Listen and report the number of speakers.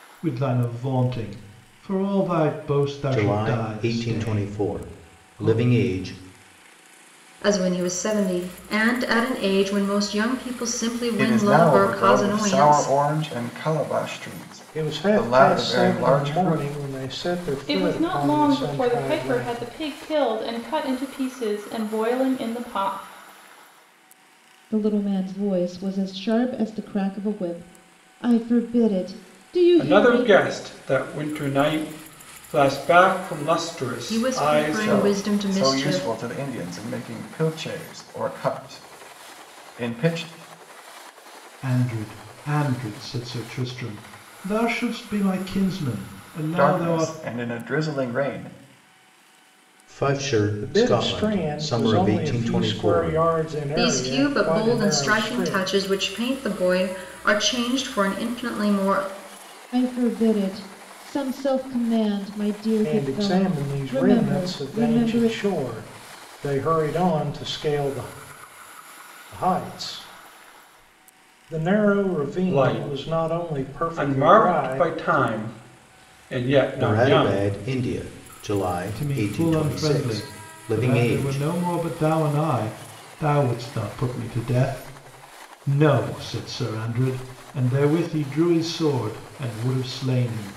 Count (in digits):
8